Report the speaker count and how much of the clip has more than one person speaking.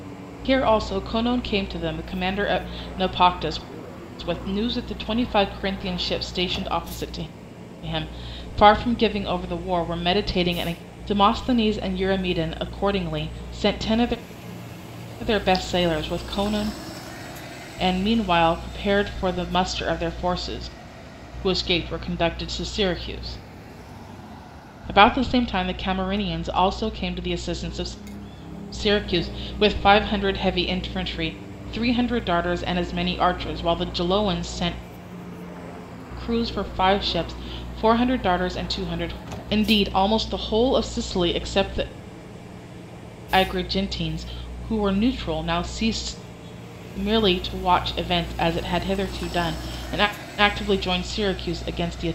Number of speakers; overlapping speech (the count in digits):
1, no overlap